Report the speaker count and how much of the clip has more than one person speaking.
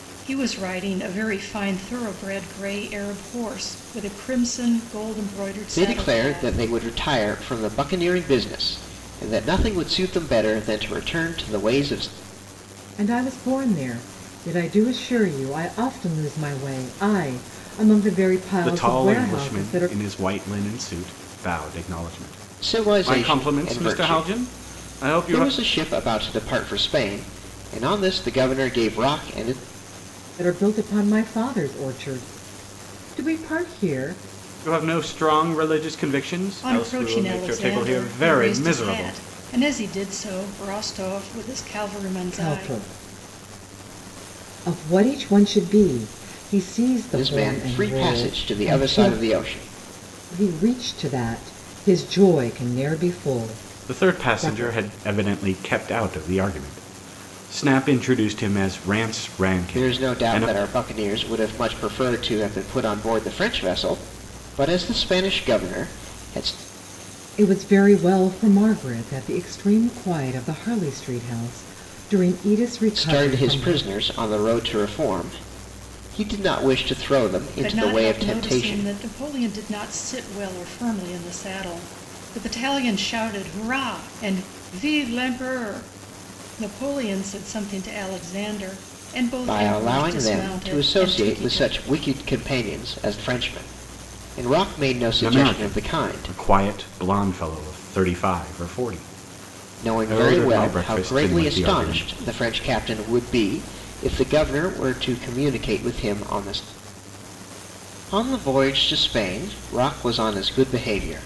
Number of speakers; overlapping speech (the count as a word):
four, about 18%